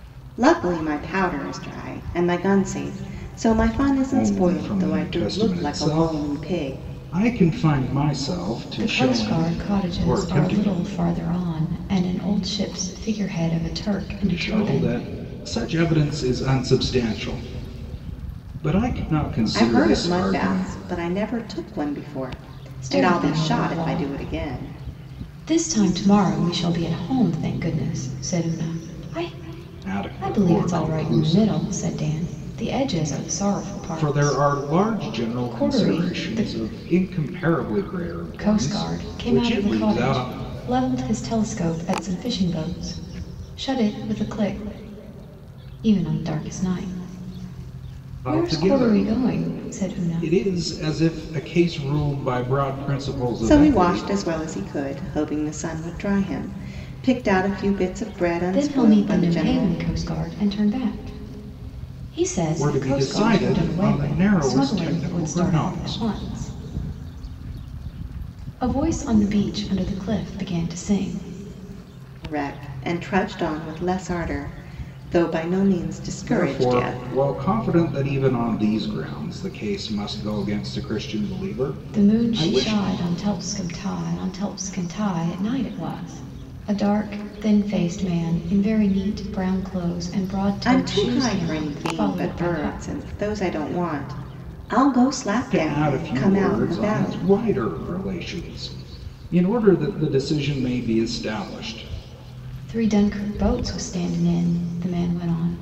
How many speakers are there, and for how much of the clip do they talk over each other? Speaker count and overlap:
3, about 27%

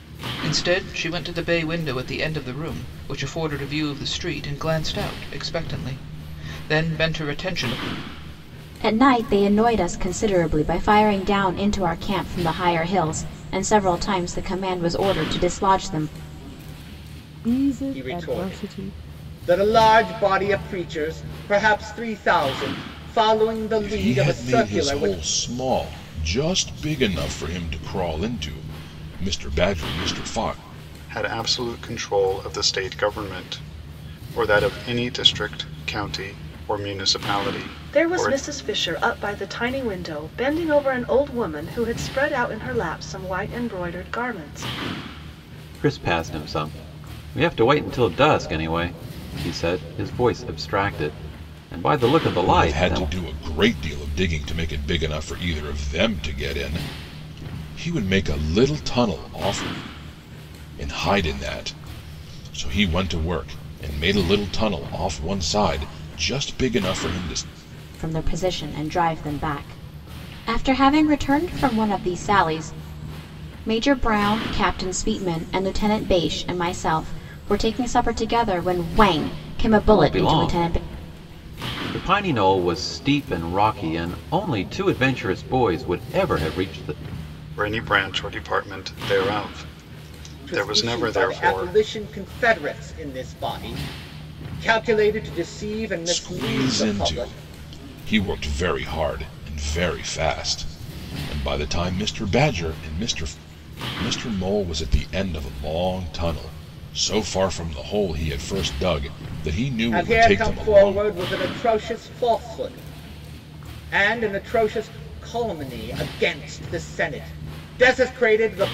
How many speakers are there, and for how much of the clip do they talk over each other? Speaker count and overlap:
8, about 7%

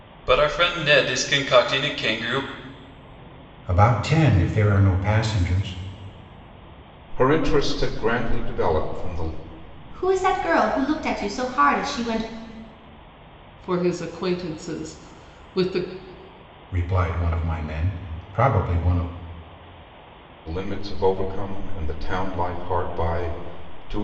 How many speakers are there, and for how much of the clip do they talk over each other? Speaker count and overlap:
5, no overlap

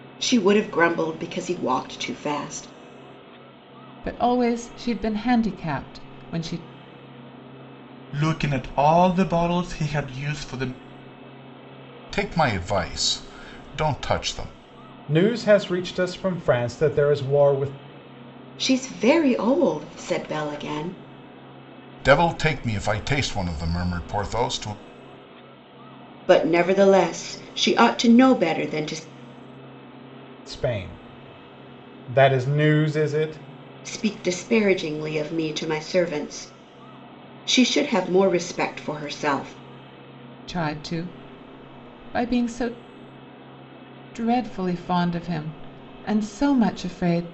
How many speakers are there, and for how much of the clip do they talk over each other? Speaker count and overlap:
5, no overlap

